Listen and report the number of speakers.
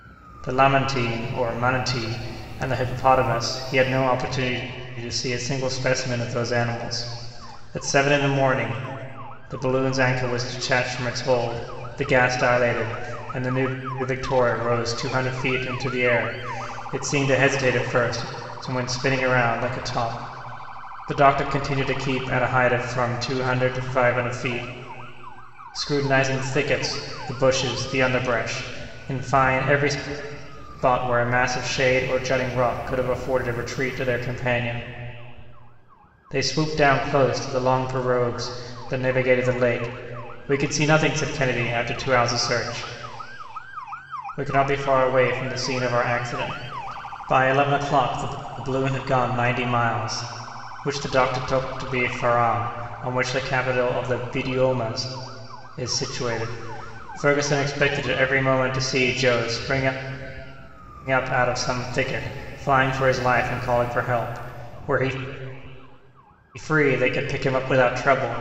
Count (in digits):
1